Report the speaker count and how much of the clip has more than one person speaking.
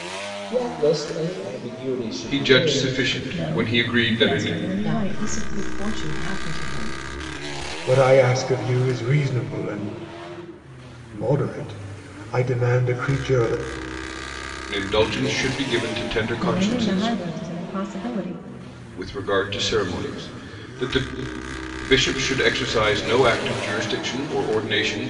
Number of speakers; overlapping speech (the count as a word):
five, about 13%